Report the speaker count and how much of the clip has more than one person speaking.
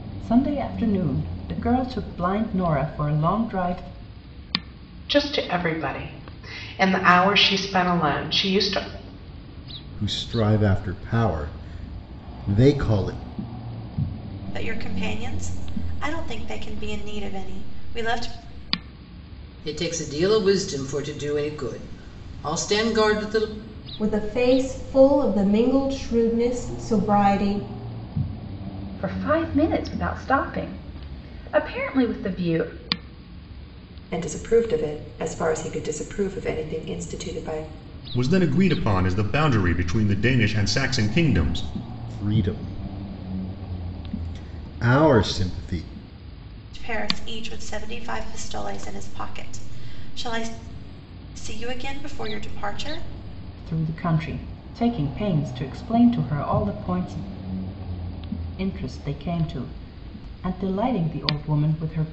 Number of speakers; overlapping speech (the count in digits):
9, no overlap